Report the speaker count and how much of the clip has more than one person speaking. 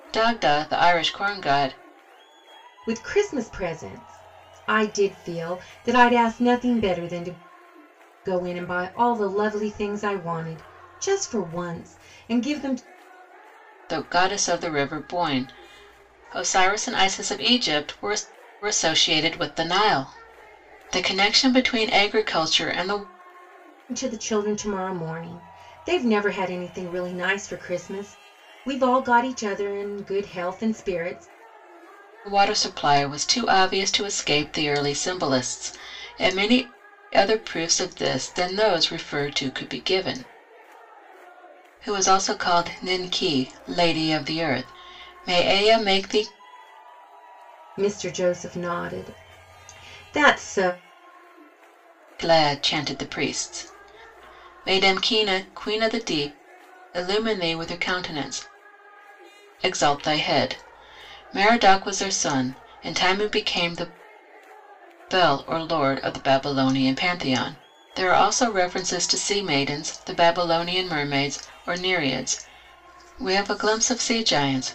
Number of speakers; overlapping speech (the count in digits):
2, no overlap